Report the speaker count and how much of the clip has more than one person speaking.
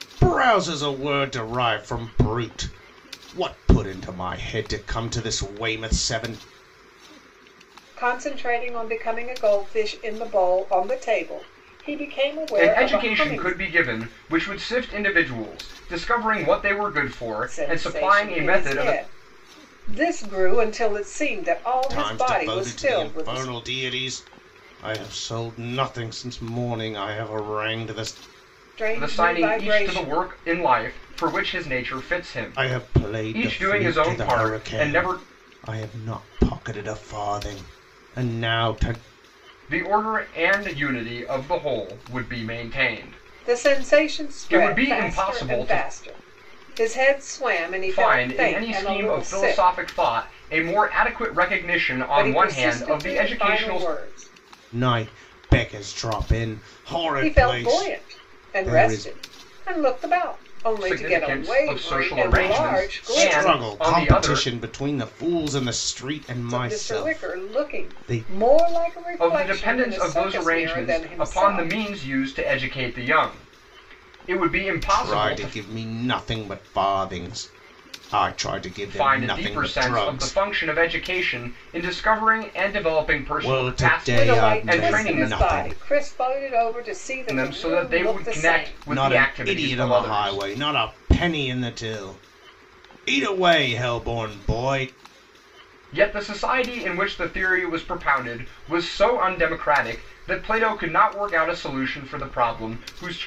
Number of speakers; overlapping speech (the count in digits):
3, about 31%